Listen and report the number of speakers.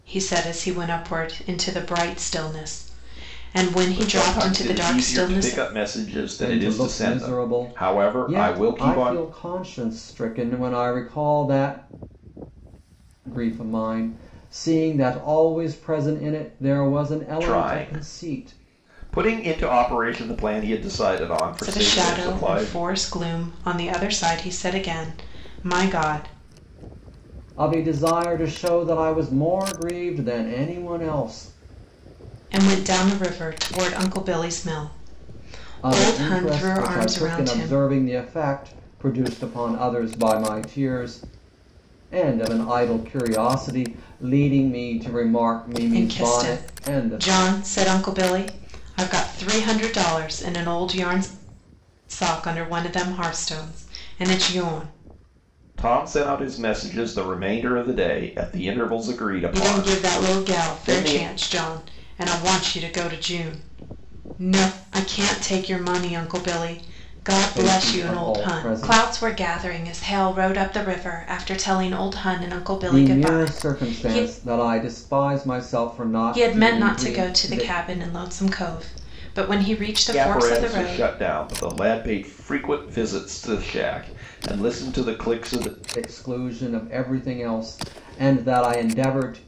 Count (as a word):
three